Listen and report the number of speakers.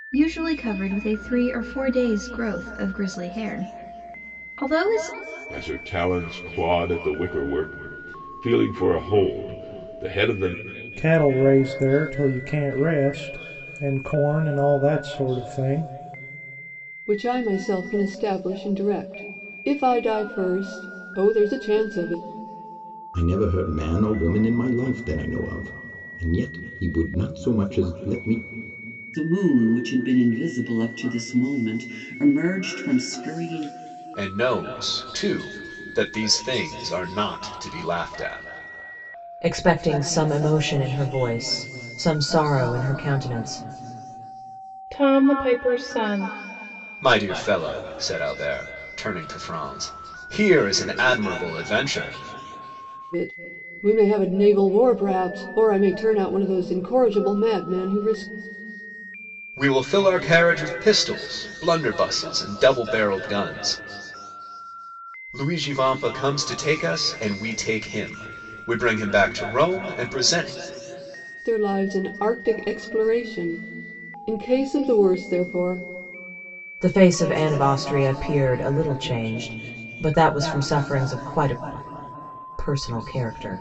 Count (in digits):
9